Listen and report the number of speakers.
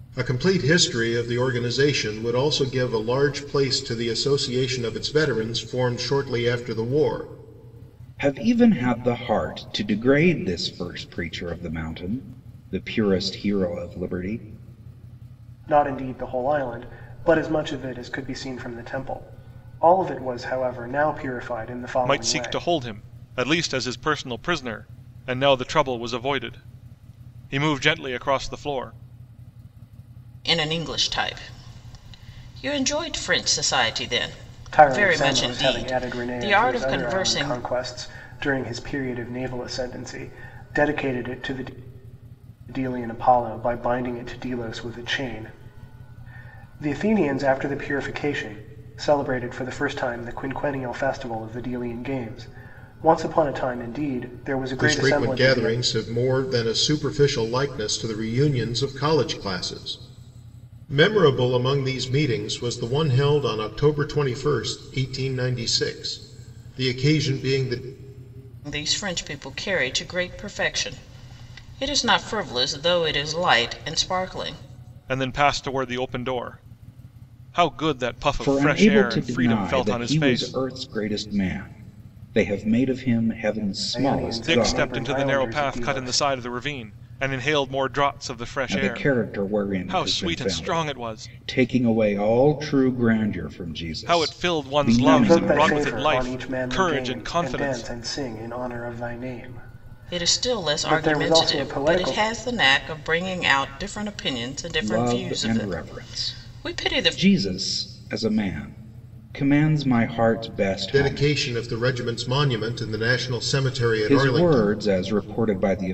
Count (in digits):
5